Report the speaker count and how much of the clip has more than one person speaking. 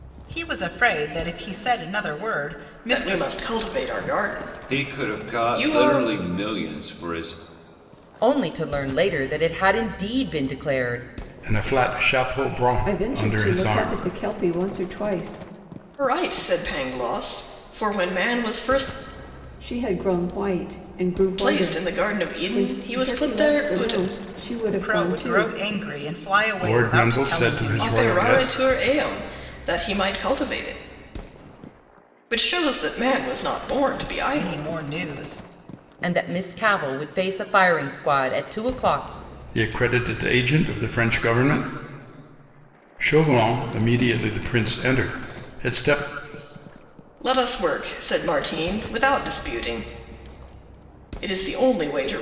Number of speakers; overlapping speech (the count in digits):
6, about 17%